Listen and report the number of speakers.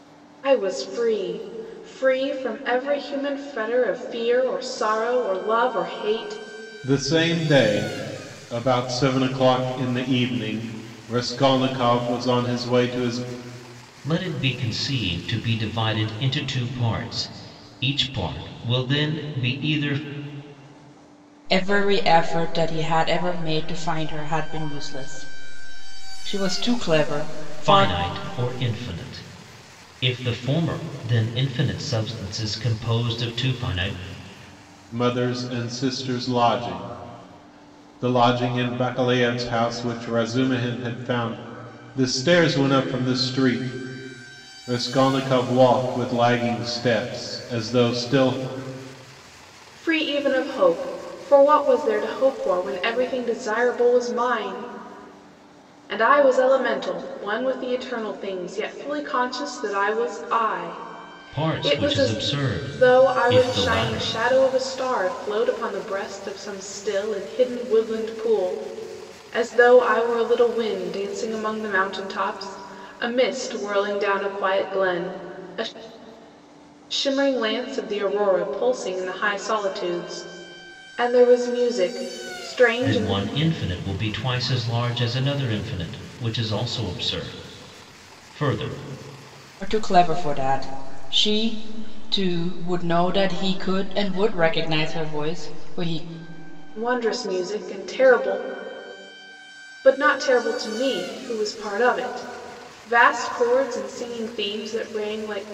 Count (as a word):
four